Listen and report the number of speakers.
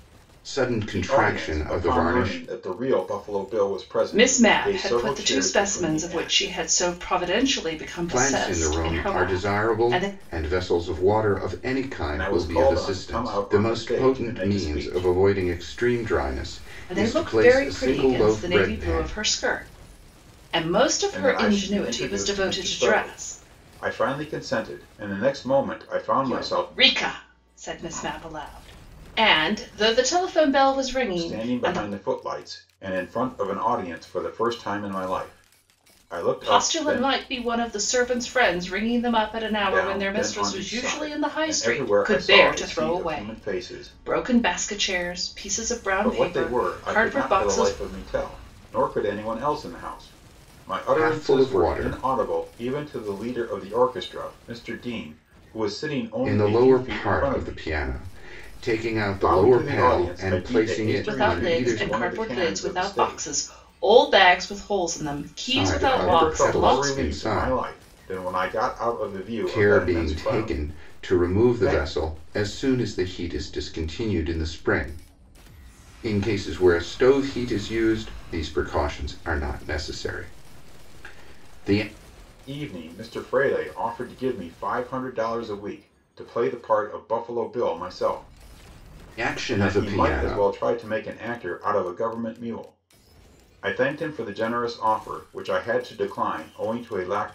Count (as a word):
three